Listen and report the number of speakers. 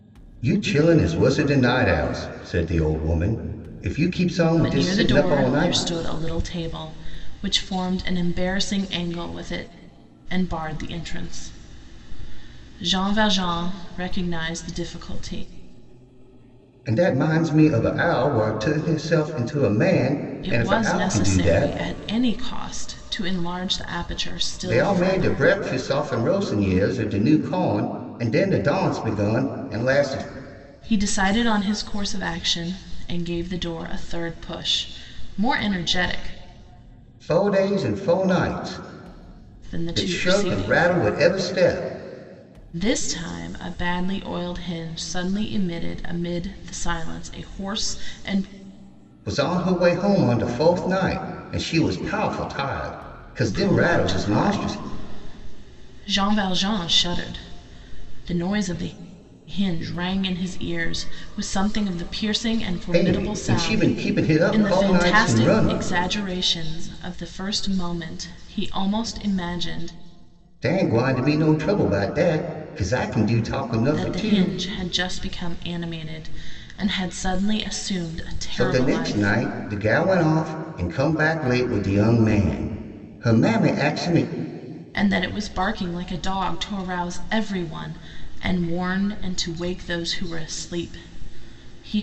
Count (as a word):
two